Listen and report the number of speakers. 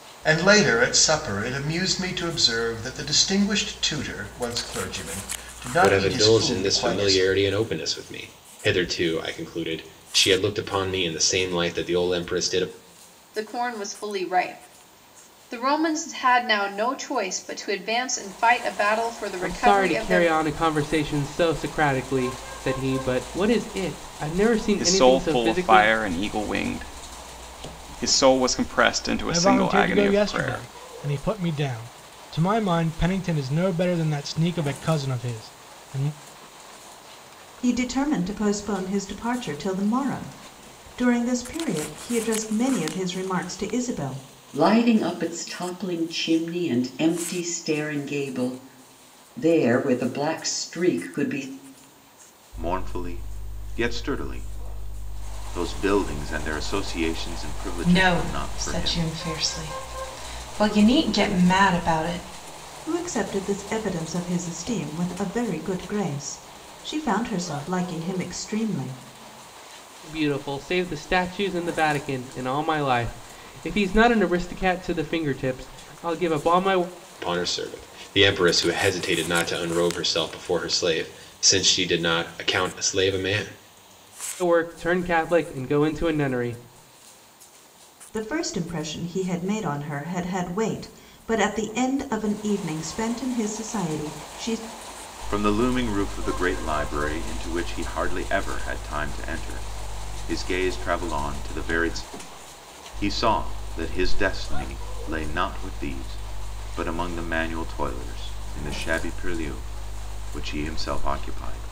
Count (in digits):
10